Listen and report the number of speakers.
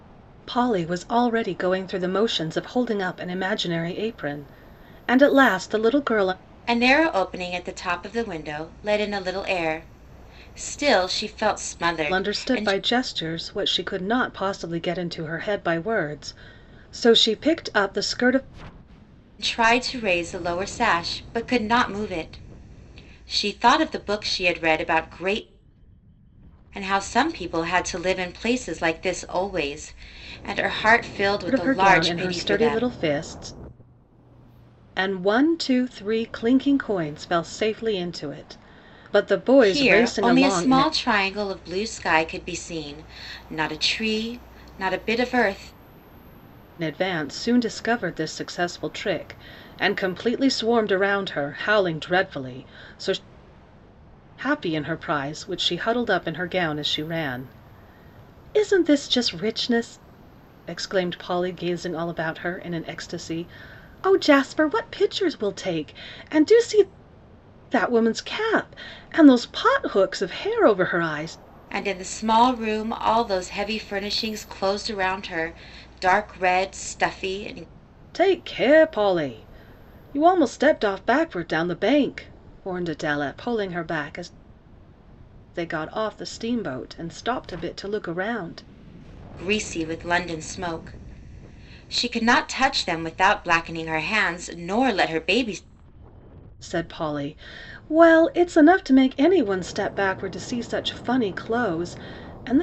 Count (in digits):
2